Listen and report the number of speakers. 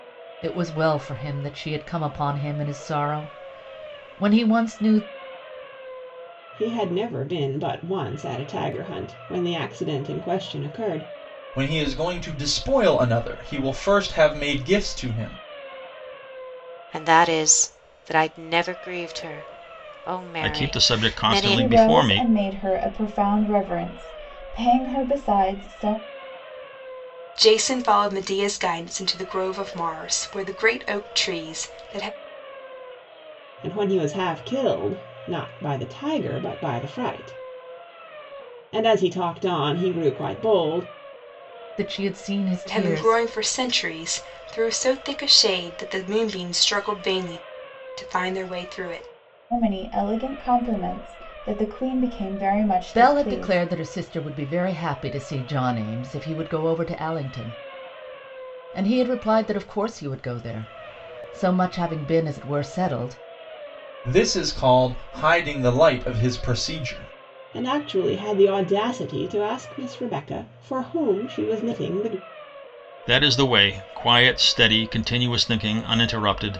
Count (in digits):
7